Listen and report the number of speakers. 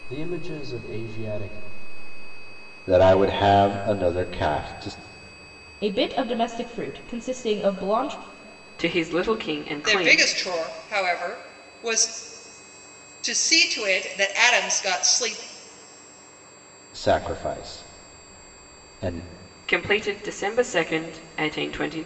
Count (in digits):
5